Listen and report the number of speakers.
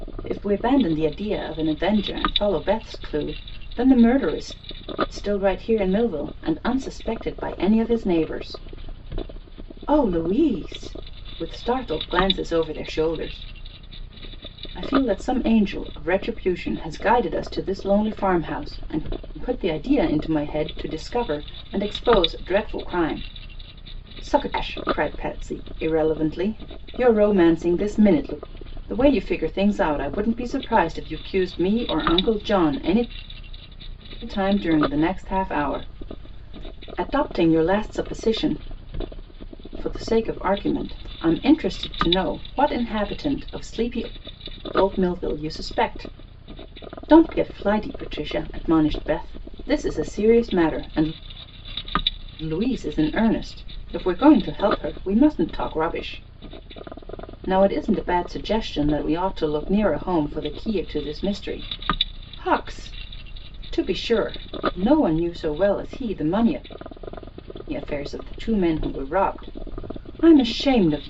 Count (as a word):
one